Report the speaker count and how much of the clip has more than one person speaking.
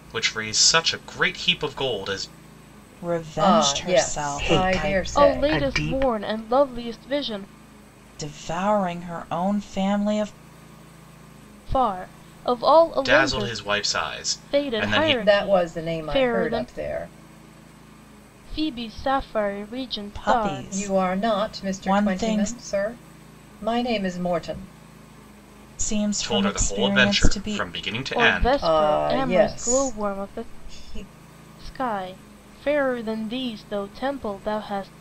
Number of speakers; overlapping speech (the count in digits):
5, about 34%